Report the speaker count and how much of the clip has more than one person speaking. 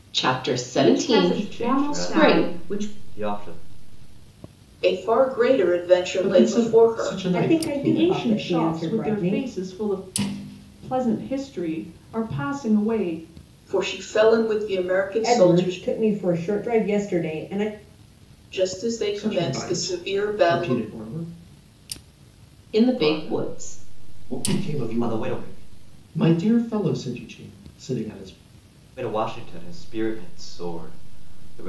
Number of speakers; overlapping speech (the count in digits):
7, about 31%